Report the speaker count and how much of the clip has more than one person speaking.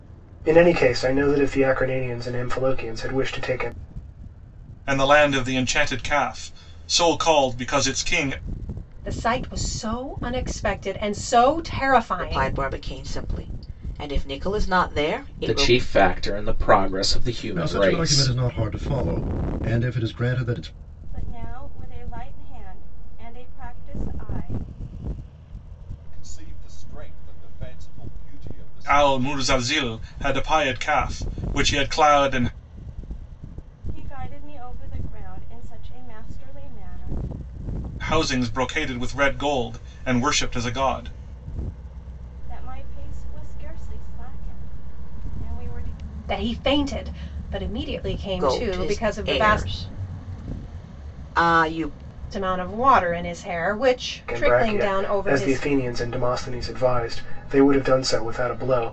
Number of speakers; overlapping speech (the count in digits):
8, about 9%